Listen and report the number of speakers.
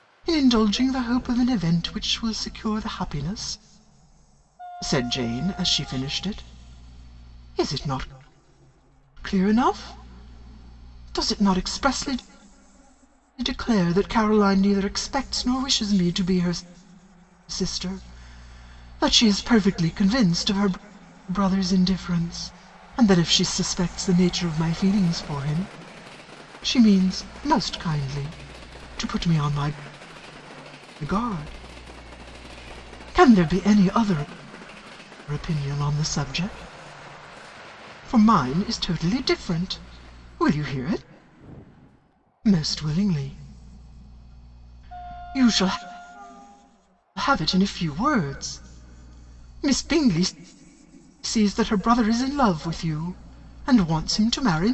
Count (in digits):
1